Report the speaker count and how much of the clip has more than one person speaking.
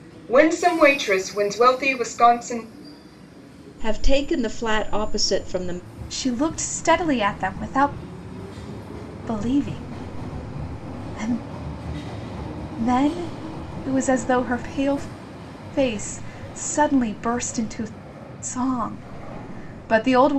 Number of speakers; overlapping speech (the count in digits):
3, no overlap